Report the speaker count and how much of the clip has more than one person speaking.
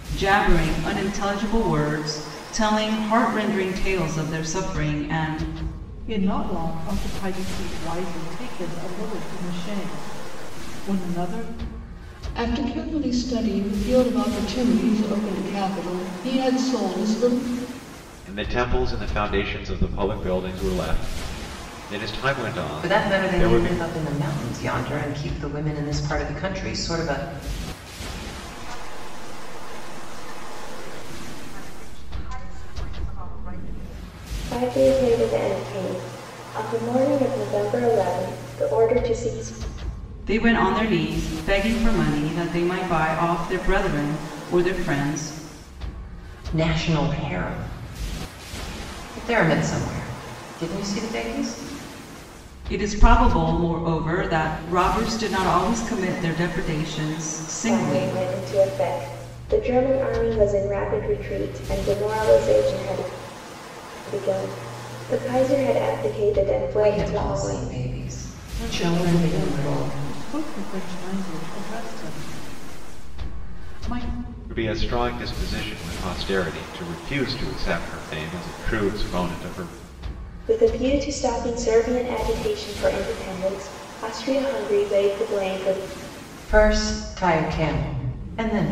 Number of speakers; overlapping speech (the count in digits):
7, about 4%